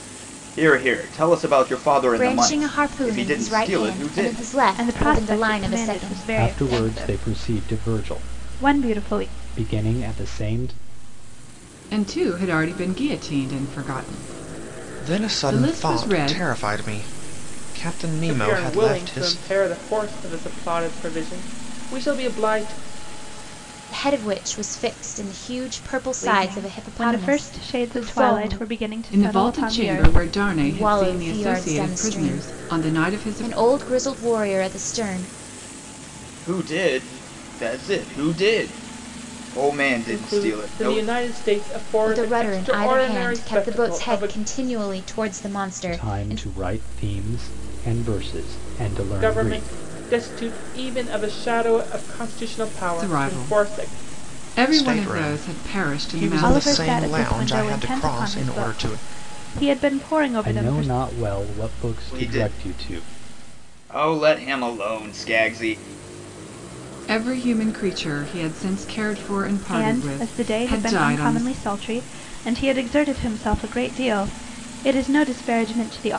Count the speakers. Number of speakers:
7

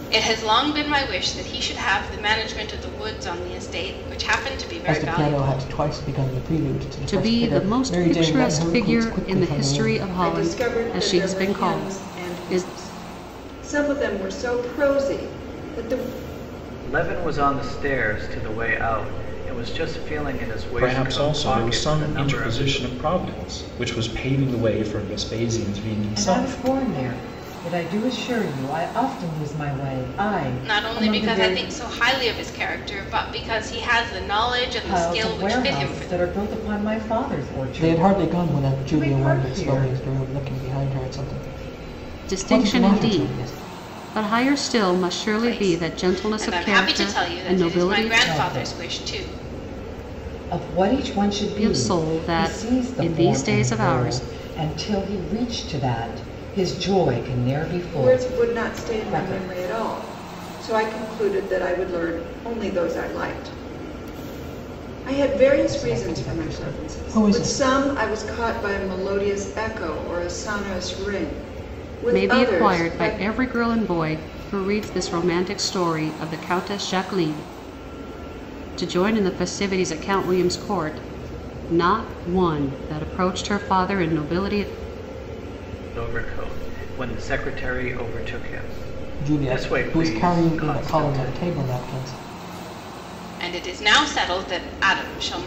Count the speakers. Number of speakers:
7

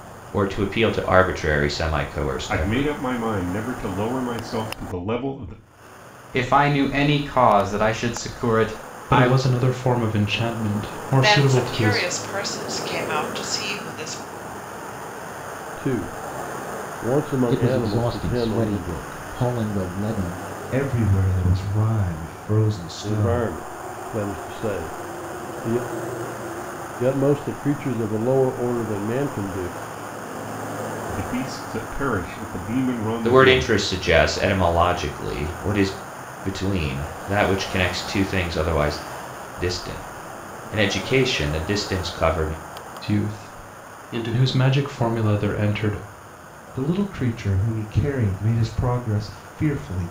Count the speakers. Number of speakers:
8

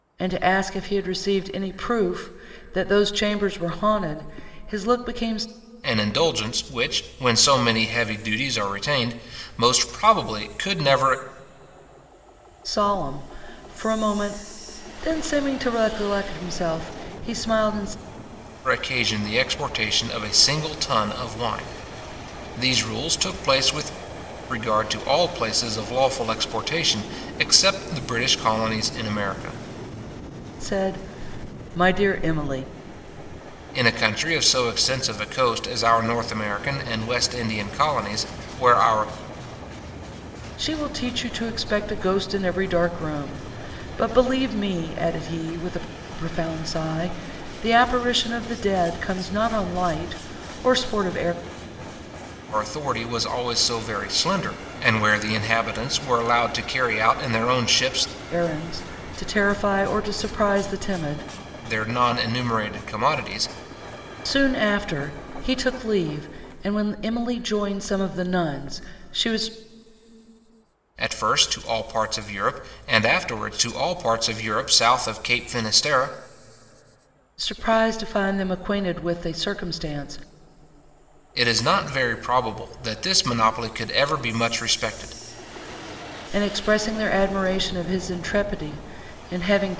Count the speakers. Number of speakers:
2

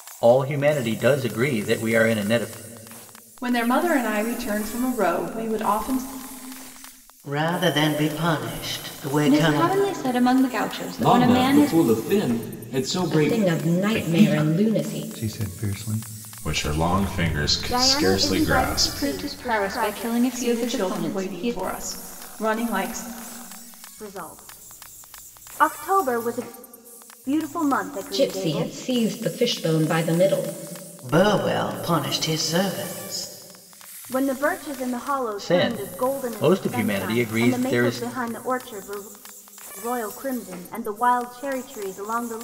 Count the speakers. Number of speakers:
9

